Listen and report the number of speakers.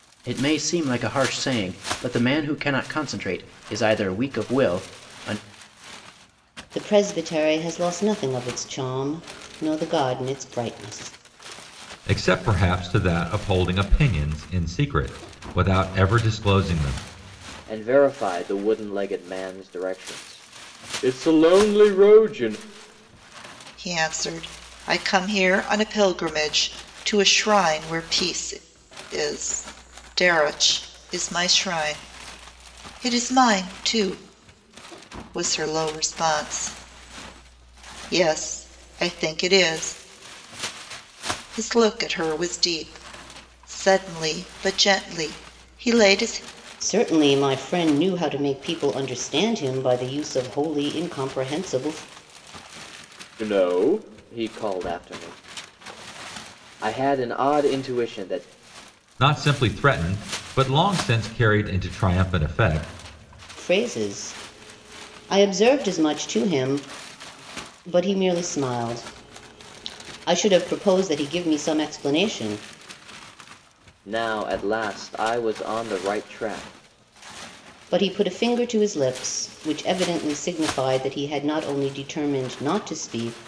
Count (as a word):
five